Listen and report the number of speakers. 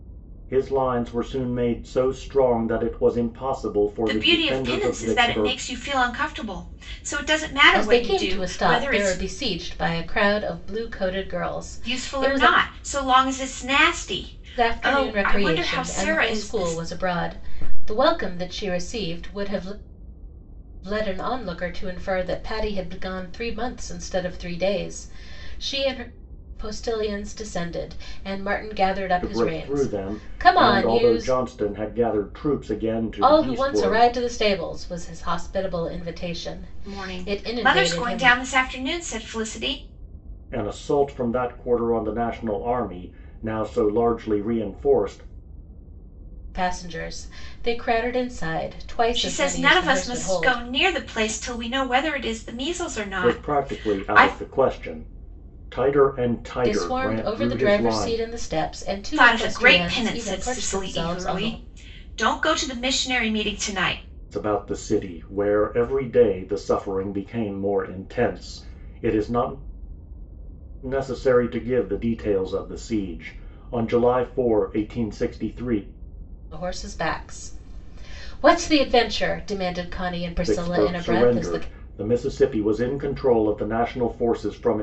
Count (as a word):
three